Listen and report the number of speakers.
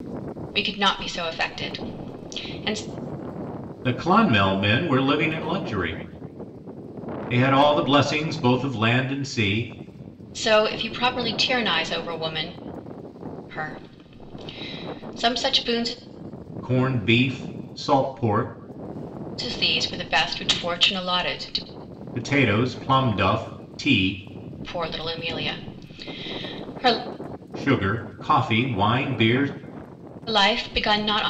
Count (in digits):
2